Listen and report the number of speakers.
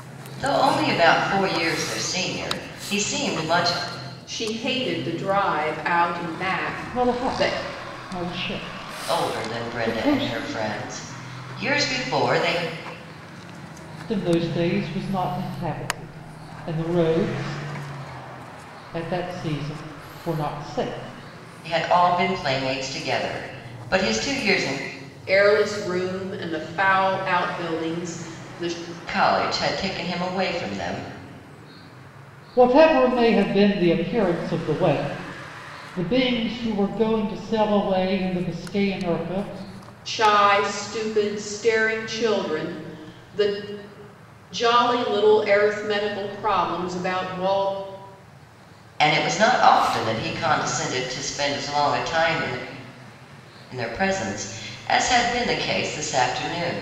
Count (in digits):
3